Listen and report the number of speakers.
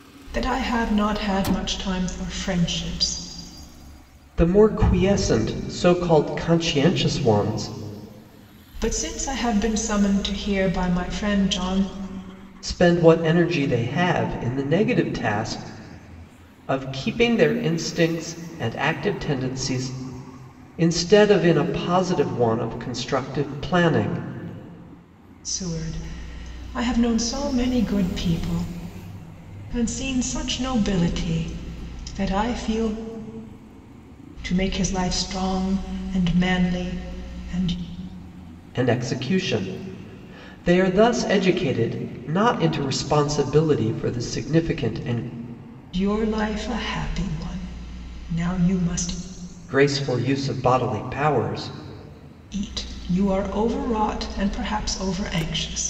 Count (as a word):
two